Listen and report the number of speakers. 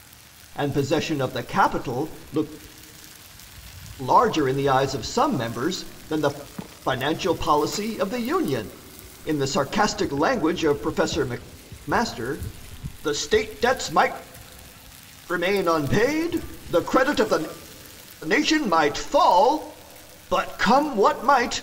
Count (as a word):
one